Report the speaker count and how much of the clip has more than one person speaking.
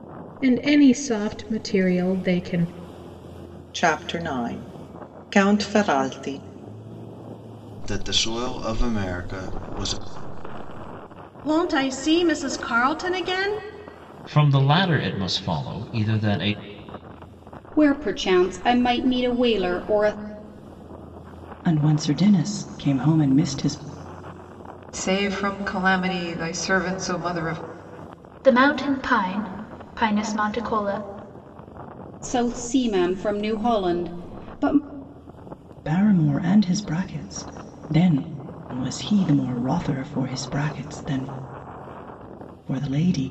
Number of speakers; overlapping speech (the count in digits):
9, no overlap